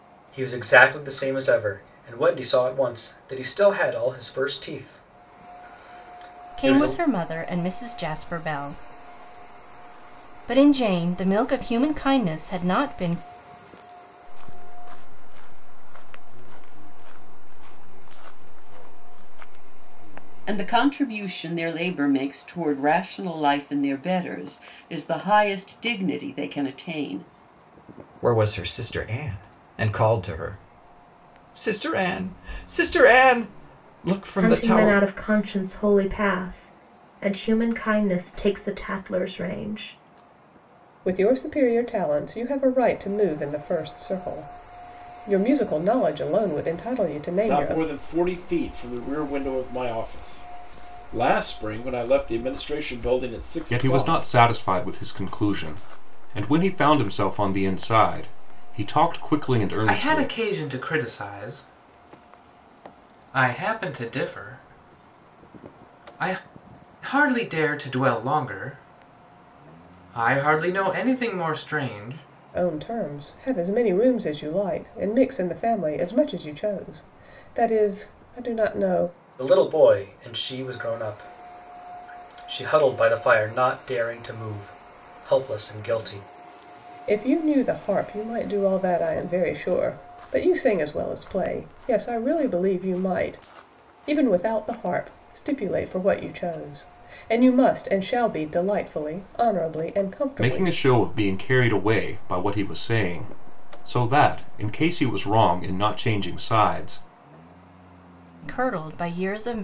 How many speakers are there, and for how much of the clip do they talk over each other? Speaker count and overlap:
10, about 3%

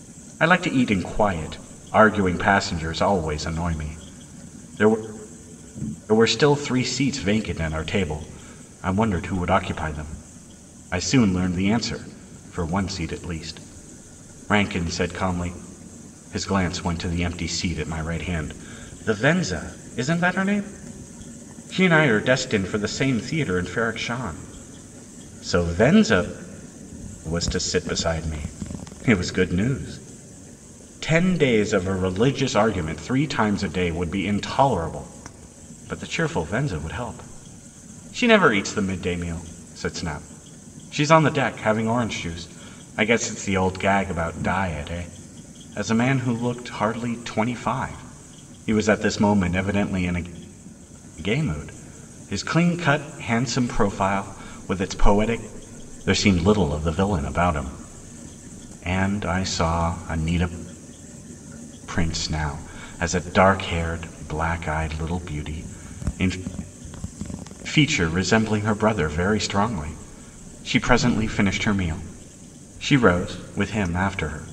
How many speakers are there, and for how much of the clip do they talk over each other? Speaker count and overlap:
1, no overlap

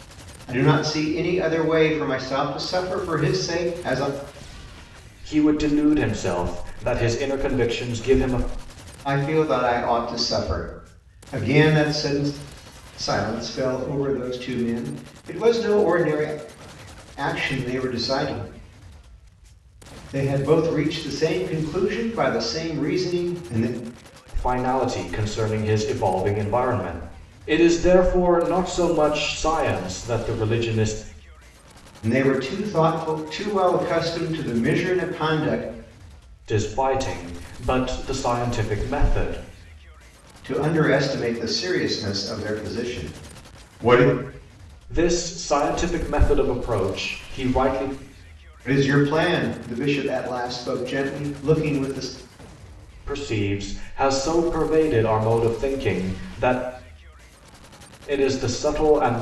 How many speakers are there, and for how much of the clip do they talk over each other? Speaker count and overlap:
2, no overlap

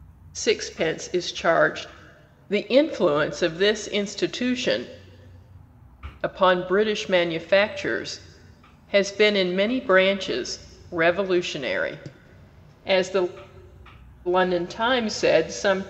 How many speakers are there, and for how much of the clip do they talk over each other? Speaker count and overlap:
1, no overlap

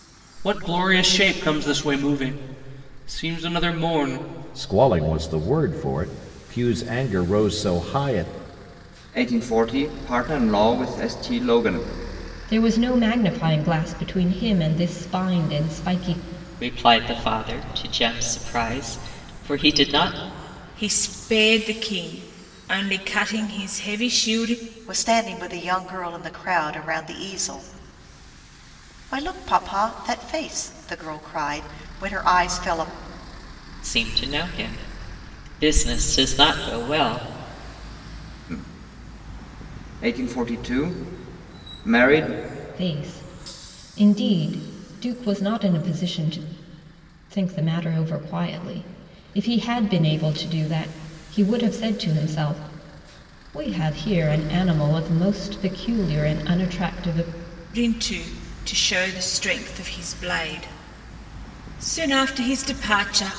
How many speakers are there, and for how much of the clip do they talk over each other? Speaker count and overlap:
7, no overlap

